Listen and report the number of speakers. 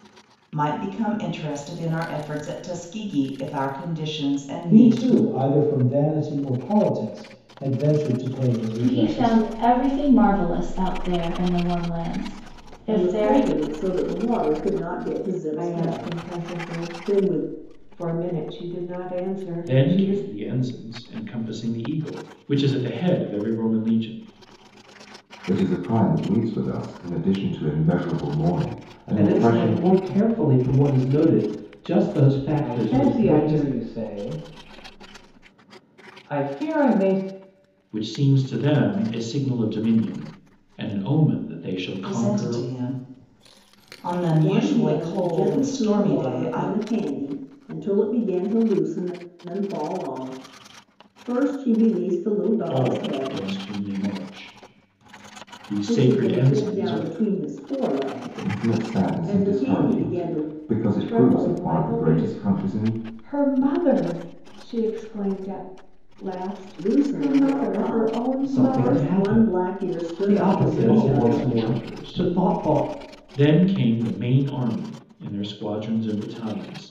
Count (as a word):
nine